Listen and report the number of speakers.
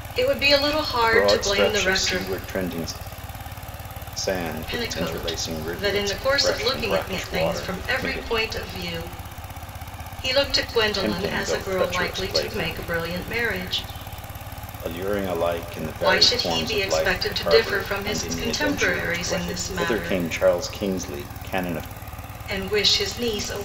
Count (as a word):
two